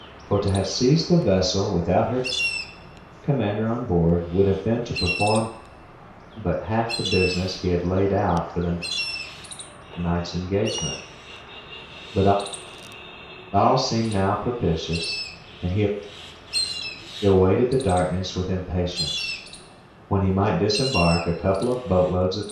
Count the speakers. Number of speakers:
1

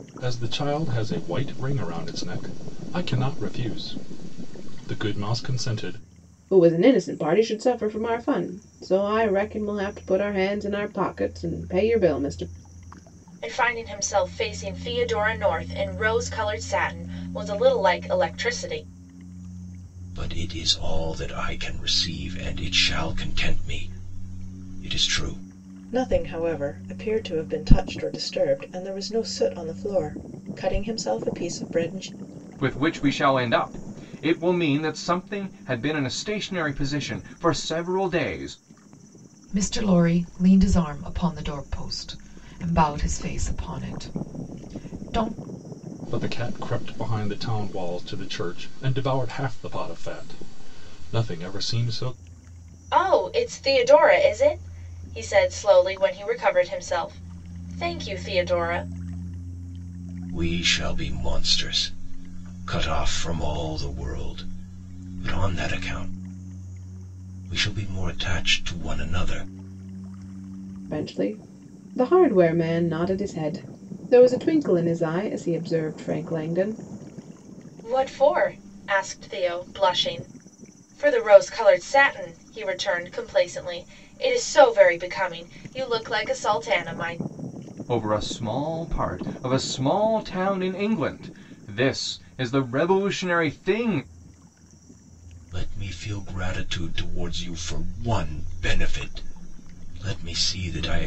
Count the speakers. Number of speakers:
7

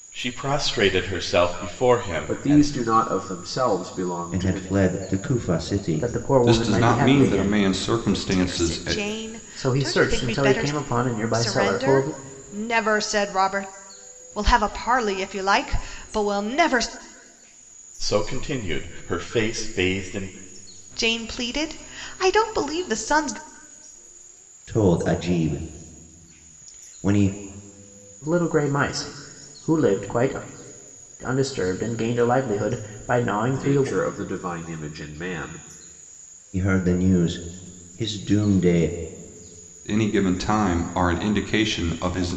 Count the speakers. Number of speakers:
6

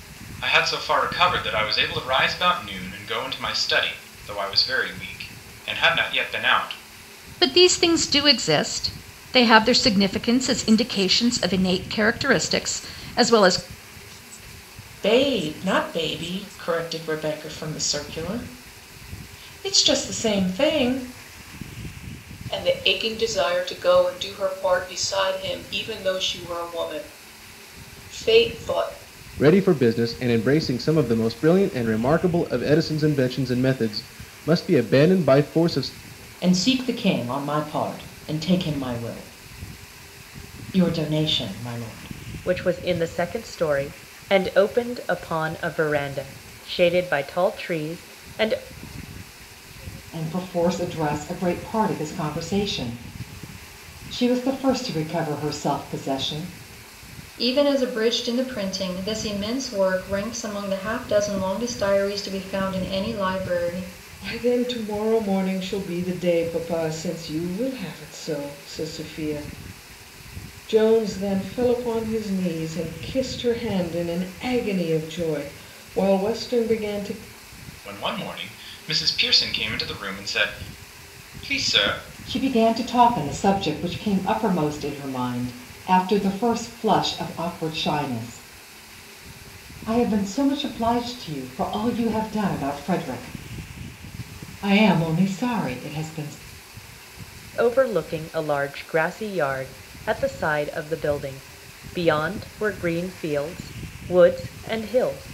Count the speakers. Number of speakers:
10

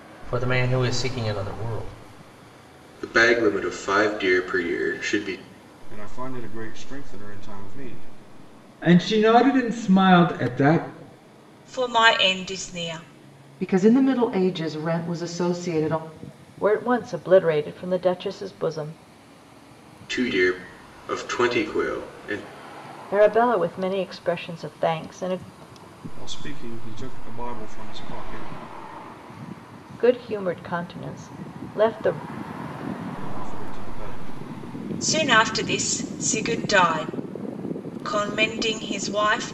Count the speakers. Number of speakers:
7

